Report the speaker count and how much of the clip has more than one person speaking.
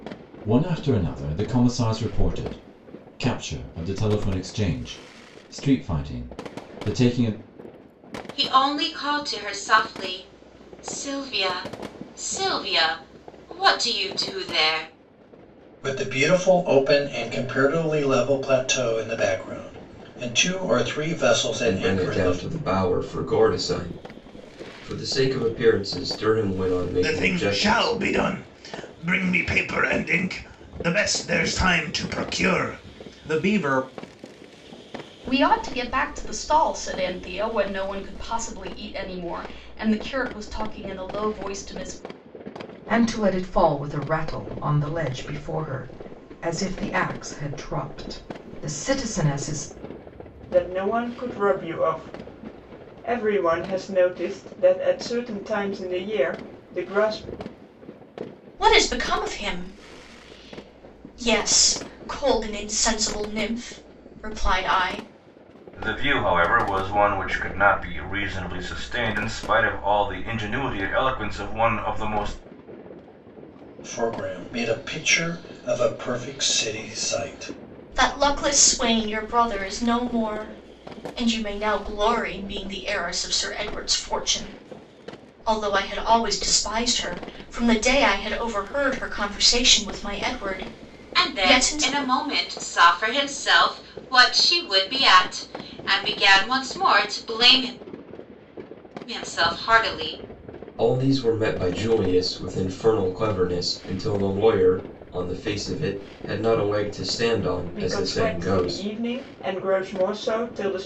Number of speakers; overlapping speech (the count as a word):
ten, about 3%